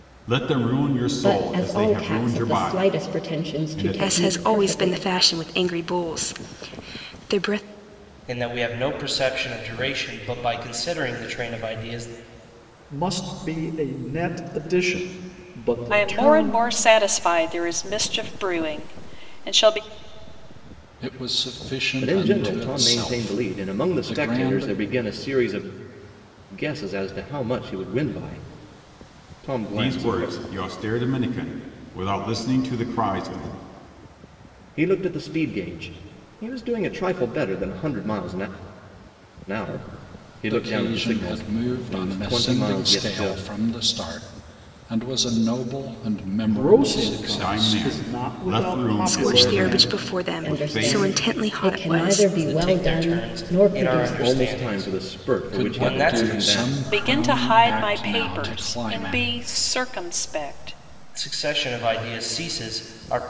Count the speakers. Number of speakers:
eight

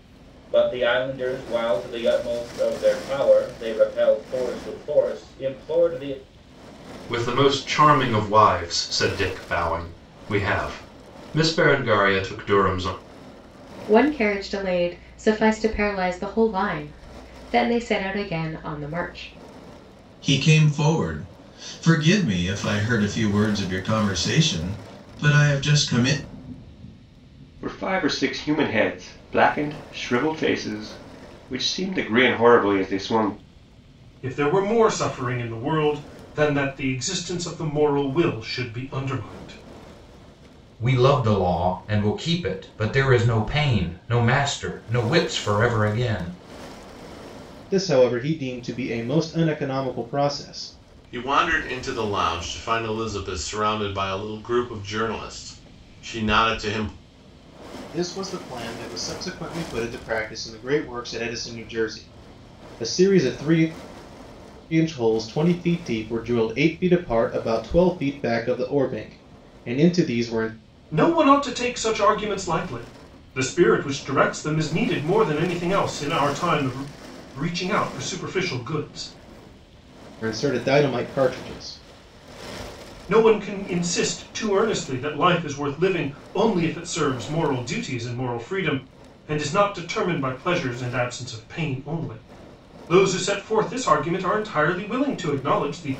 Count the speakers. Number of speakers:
nine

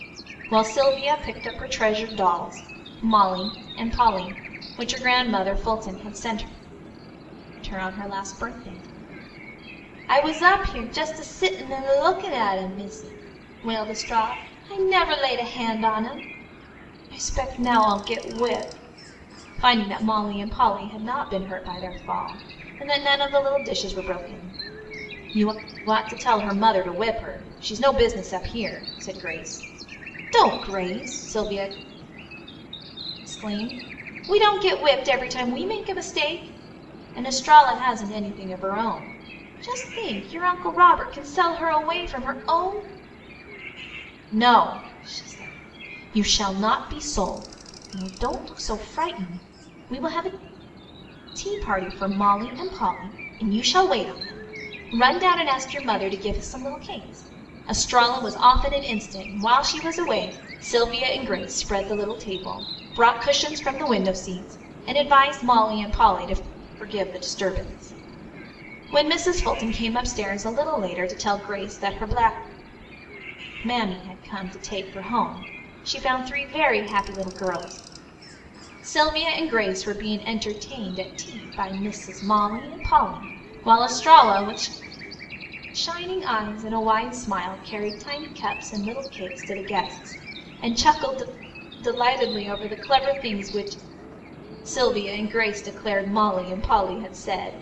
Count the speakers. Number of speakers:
one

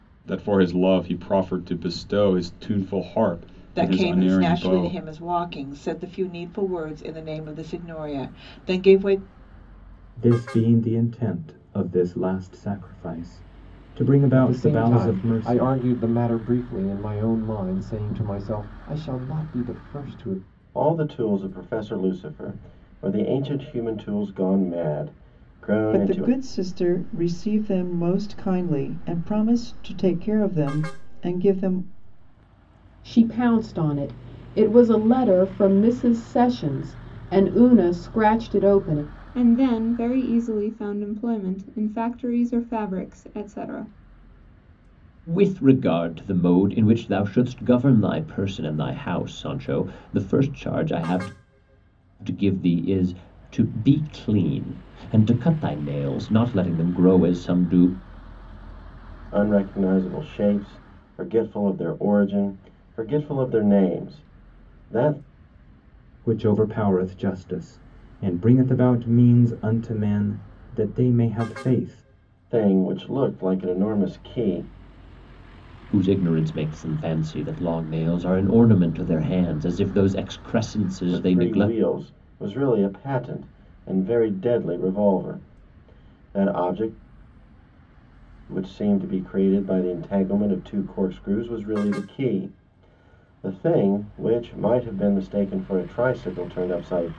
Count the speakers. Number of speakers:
nine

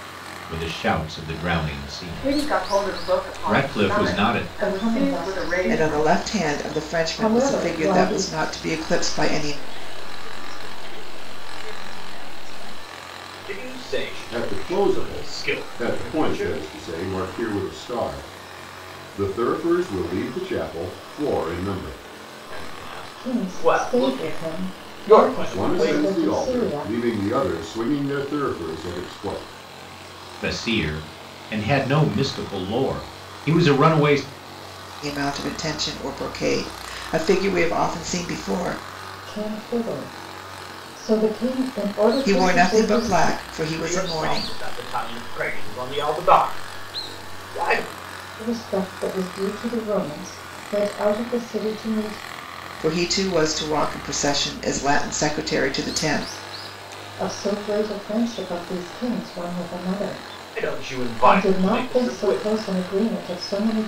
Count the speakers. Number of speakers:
seven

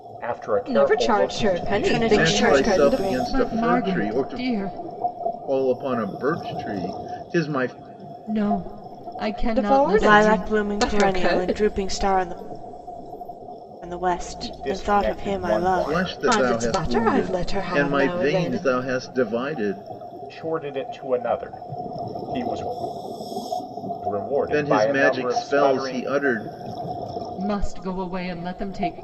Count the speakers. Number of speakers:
five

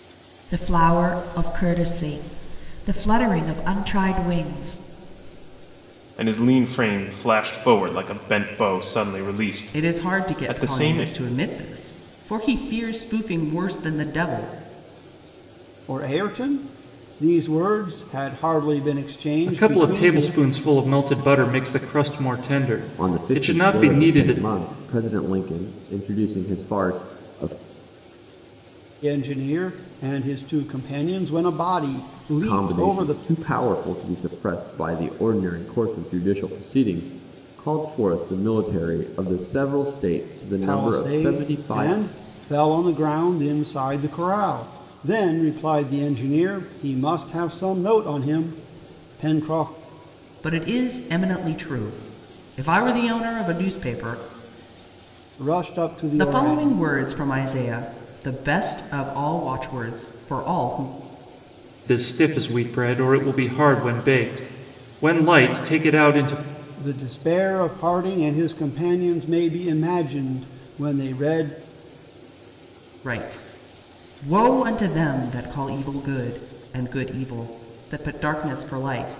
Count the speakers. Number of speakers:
six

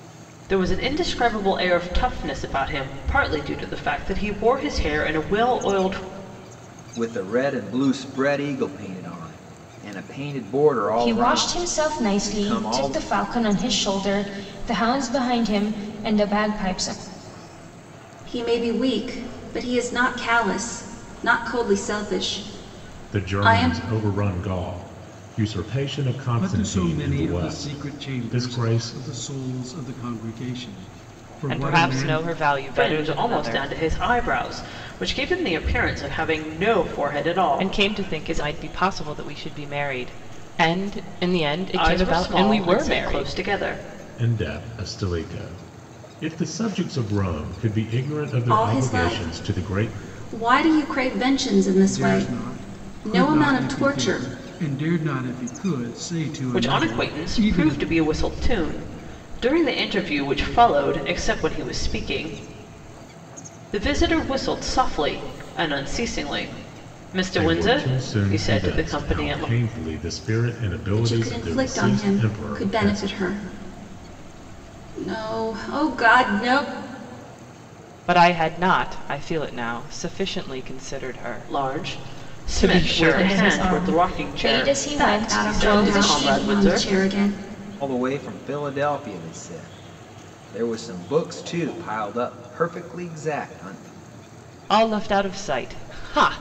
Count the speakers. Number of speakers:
seven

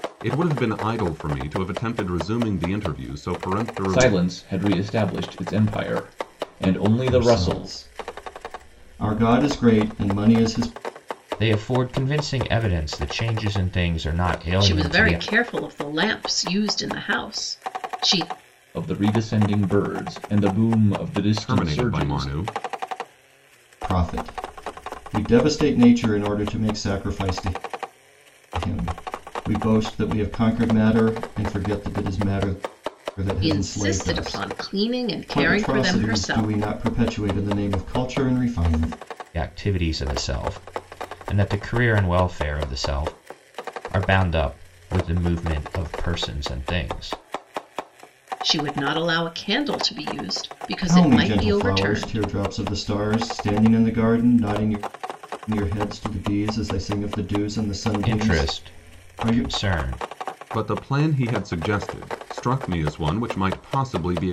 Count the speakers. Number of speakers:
five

